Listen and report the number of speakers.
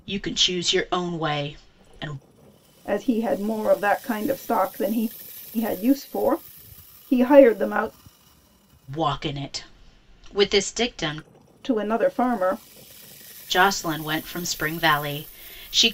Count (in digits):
2